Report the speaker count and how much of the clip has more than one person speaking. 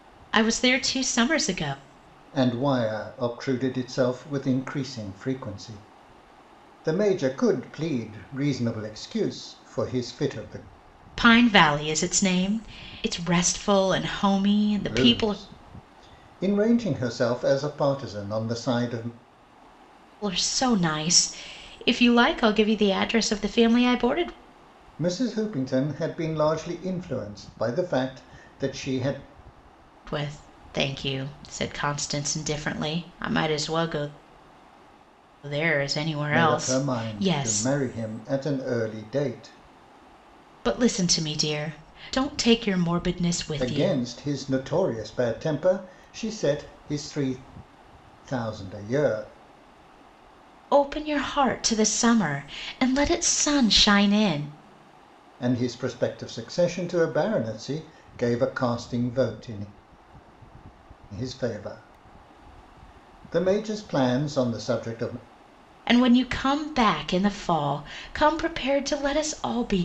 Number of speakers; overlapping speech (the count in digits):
2, about 3%